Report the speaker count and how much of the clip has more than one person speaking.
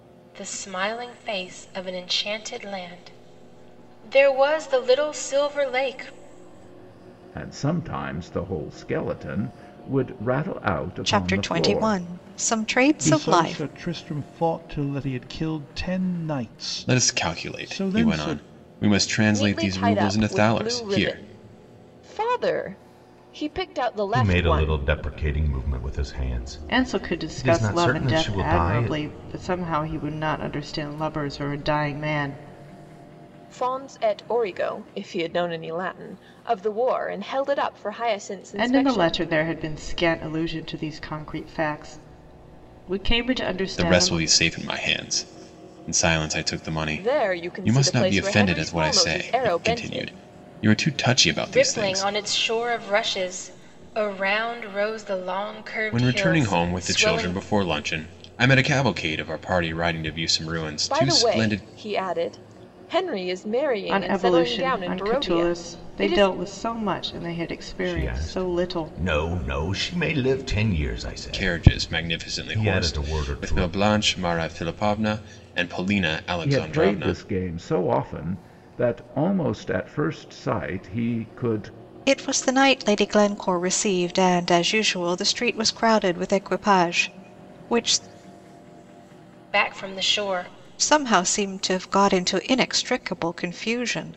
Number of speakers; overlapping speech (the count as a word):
eight, about 25%